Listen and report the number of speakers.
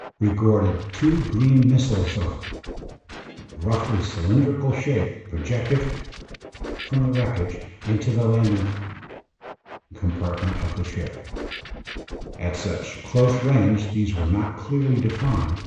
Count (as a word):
one